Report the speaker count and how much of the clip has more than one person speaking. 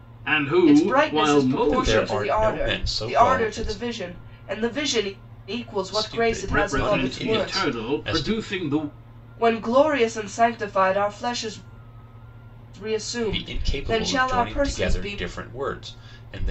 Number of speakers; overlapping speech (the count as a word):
three, about 44%